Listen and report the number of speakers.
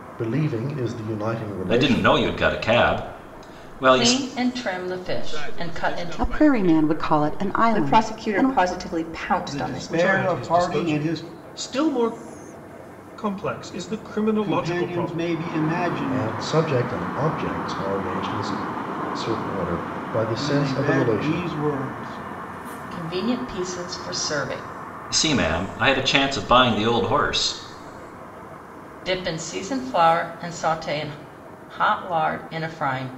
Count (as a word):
eight